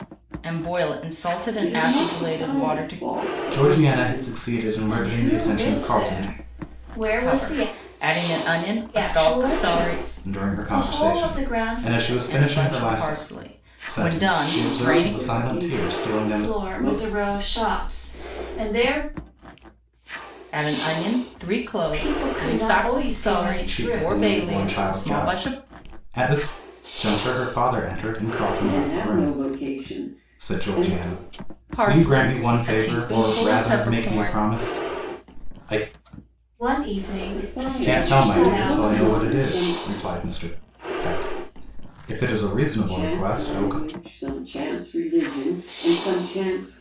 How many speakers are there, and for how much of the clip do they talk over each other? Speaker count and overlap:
four, about 48%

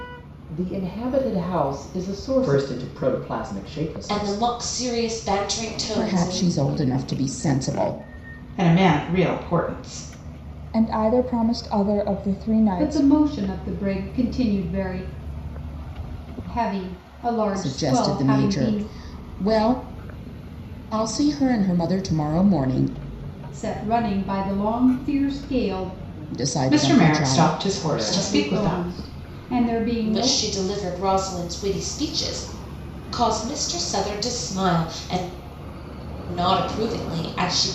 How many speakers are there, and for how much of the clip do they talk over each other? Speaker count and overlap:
seven, about 15%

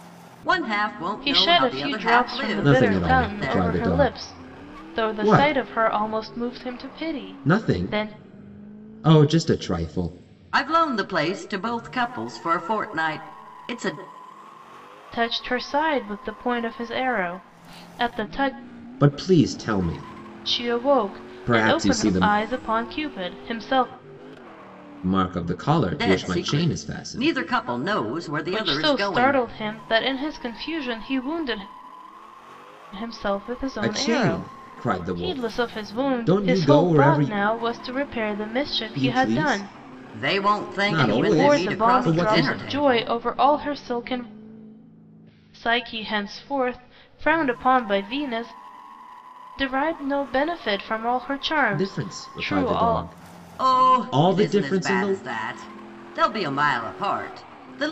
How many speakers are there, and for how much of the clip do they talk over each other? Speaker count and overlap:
three, about 33%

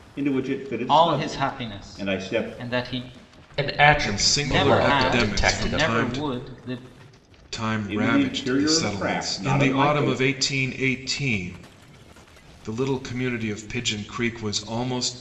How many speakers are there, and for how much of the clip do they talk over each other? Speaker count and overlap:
four, about 42%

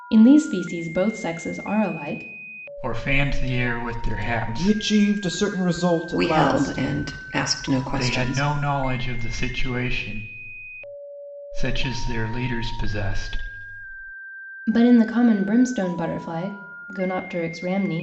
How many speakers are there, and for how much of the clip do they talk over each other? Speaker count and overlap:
four, about 9%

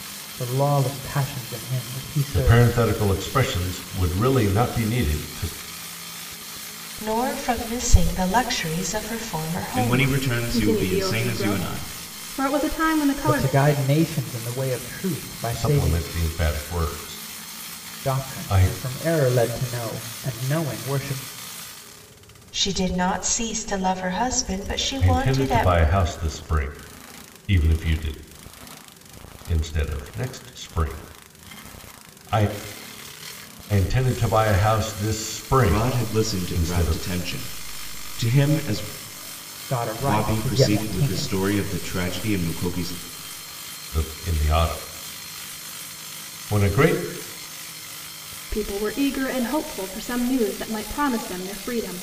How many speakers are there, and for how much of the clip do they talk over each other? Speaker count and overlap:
five, about 15%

